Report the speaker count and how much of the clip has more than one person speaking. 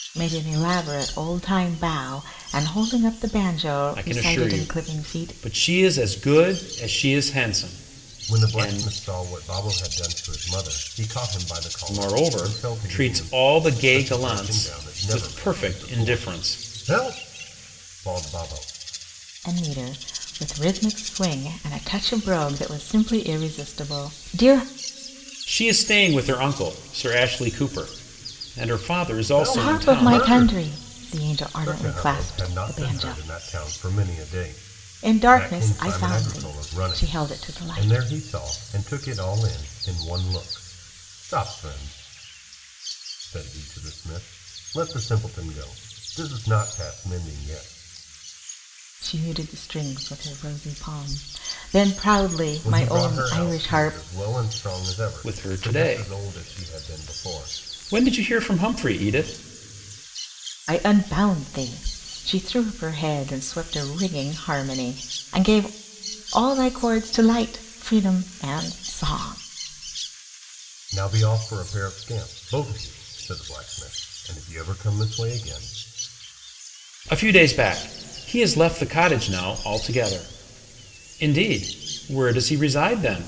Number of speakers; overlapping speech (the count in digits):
3, about 19%